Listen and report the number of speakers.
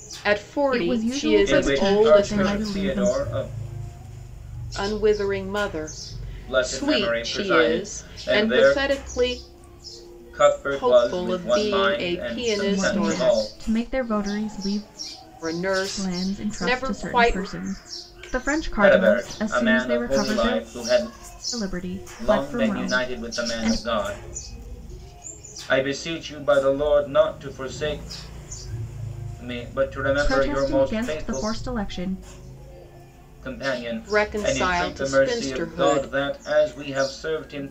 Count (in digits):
3